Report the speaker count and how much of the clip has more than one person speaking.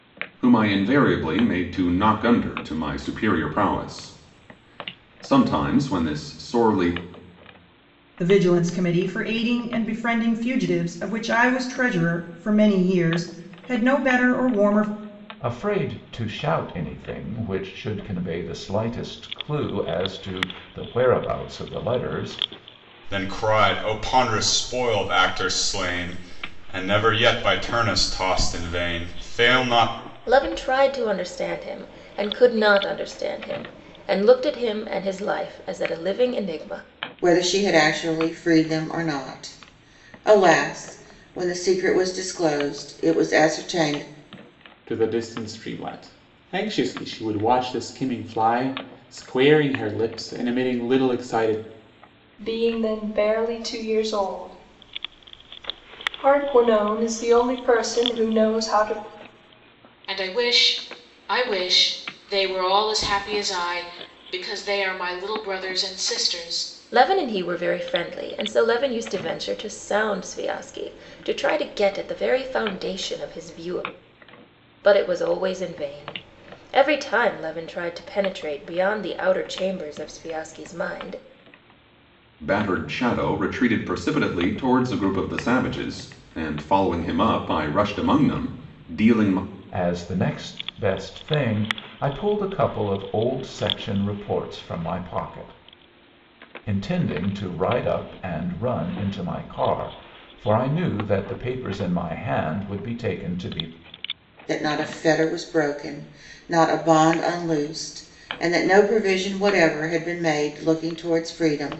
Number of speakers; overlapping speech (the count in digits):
9, no overlap